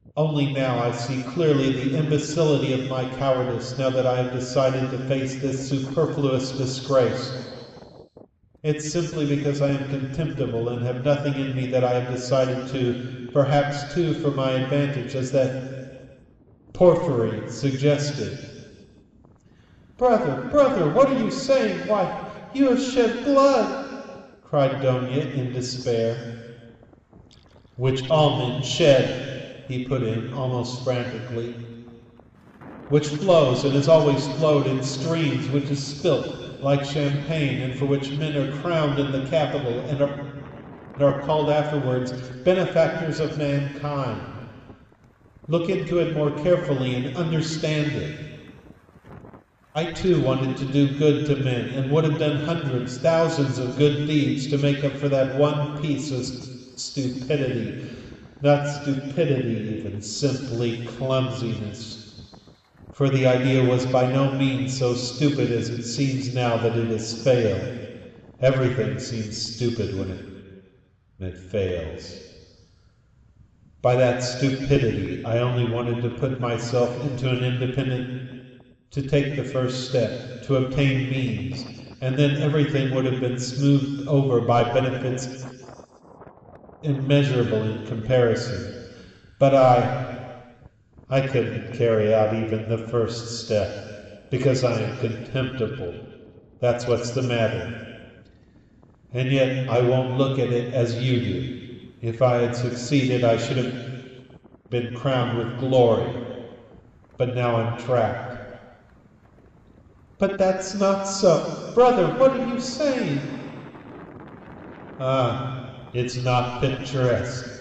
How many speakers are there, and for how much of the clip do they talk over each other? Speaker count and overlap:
1, no overlap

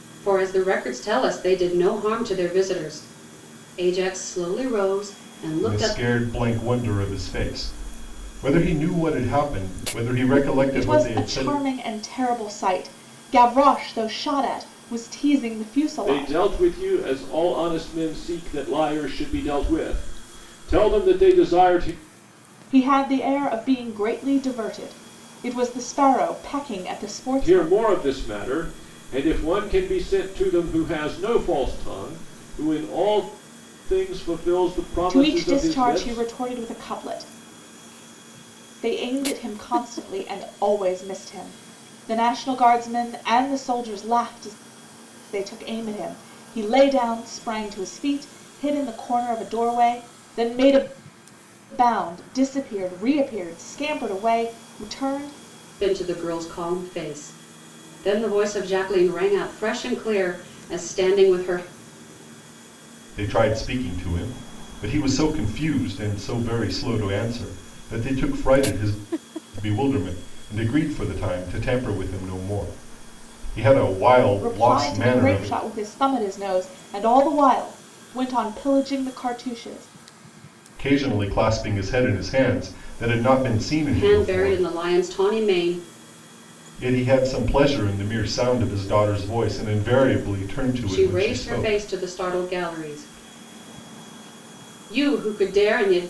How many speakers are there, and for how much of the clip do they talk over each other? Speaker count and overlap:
4, about 7%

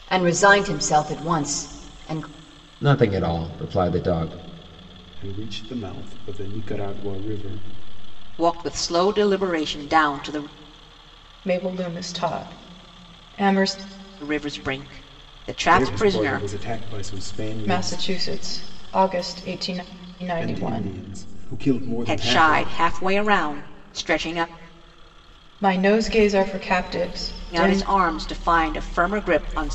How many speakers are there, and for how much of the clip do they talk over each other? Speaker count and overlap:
5, about 9%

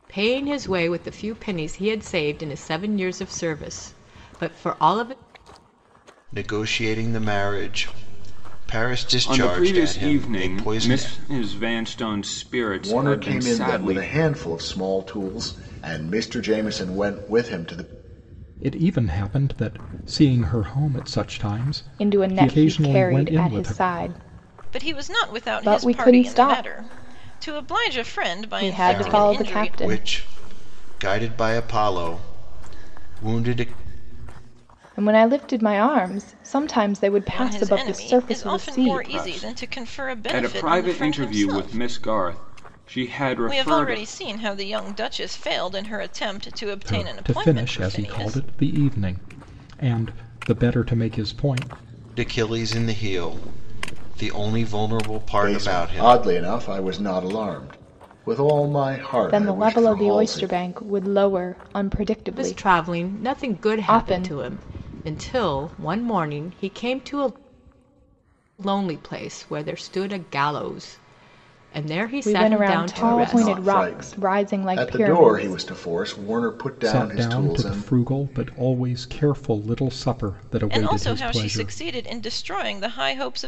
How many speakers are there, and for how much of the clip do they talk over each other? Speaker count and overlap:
7, about 30%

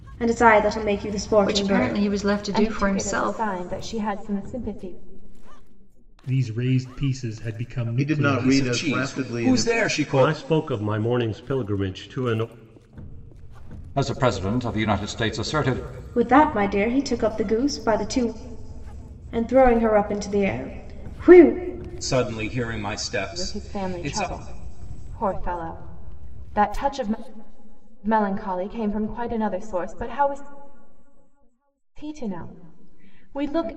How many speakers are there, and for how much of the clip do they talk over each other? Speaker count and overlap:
8, about 14%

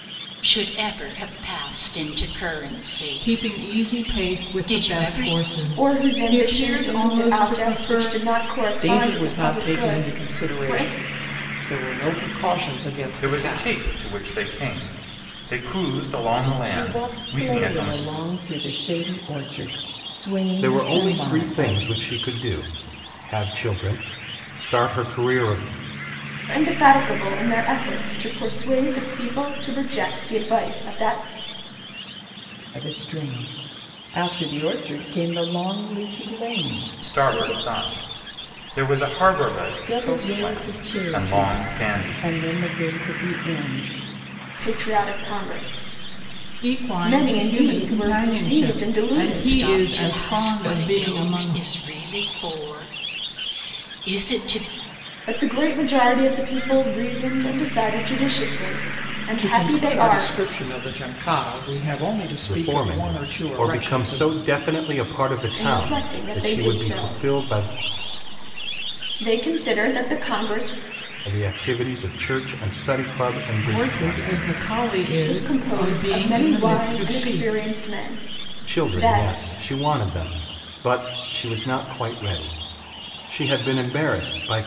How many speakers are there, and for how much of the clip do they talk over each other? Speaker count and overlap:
7, about 32%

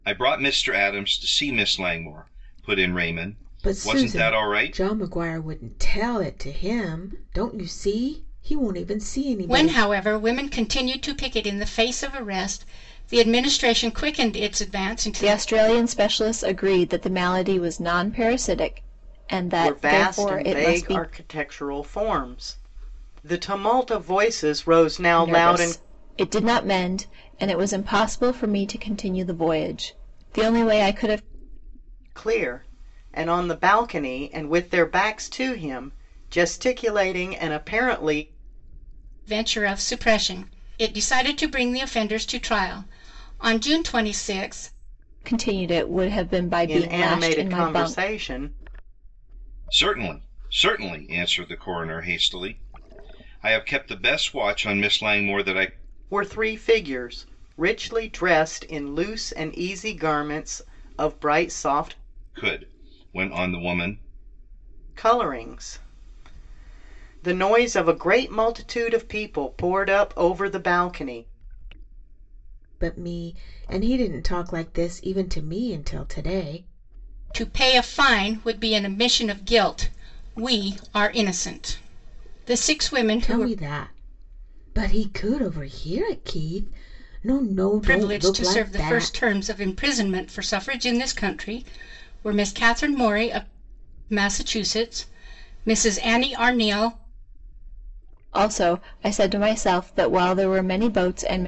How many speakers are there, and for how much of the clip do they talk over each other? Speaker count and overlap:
5, about 7%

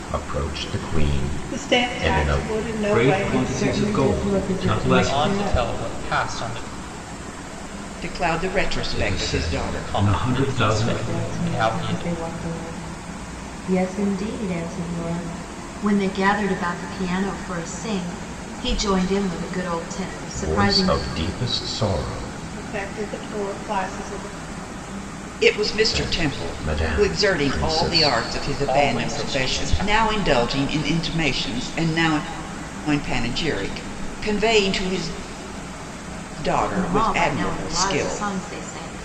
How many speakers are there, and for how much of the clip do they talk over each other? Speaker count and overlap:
6, about 33%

